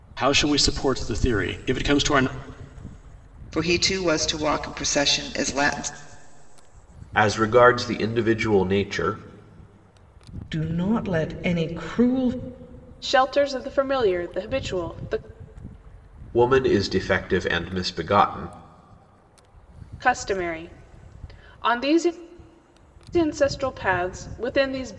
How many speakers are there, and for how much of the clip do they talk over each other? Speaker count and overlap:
5, no overlap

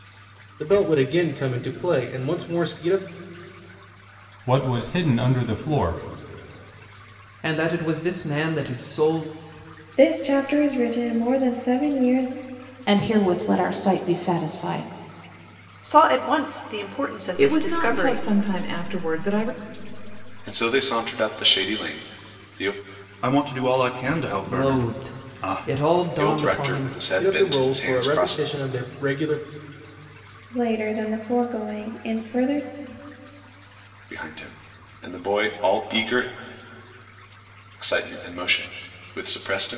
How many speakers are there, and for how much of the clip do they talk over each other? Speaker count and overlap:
9, about 10%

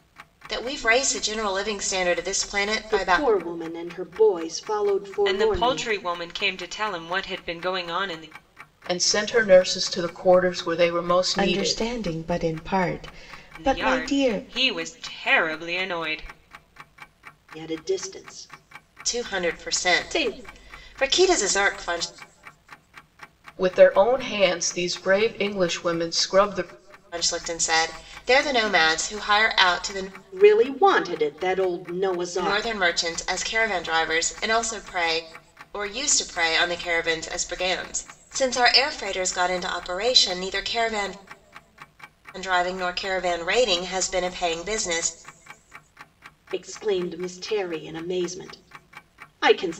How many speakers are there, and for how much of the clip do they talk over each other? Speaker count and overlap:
5, about 9%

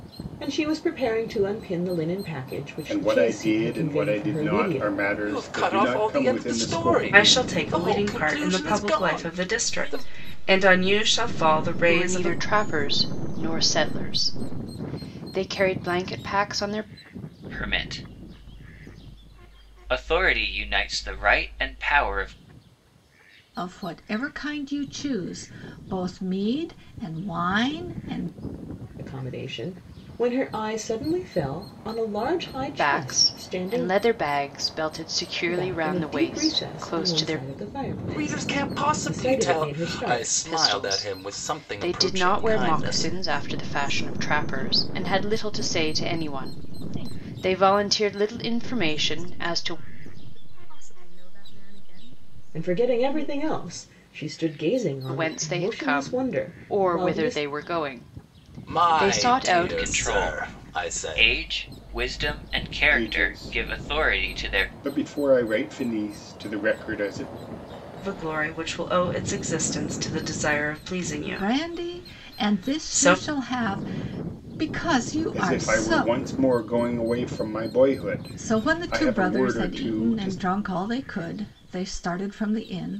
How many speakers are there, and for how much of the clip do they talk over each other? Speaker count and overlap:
8, about 46%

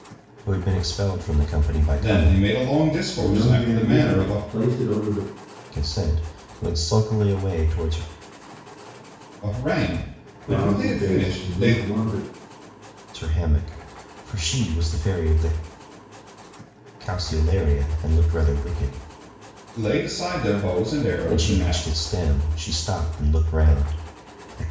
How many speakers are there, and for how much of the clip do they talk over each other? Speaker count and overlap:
3, about 16%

